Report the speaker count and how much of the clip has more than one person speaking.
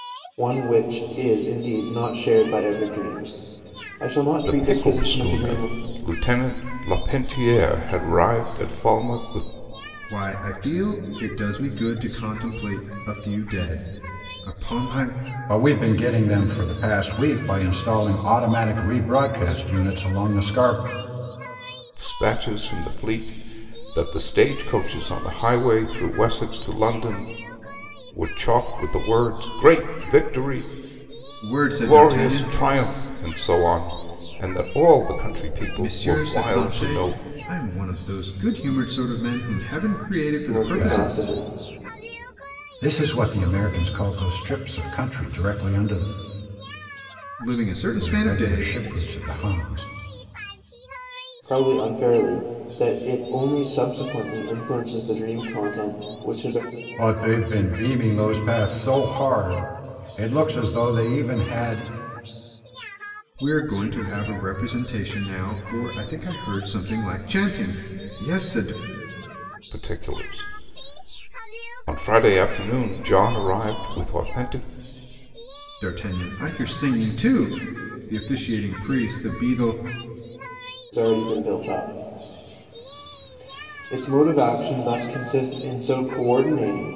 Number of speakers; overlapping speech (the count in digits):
4, about 6%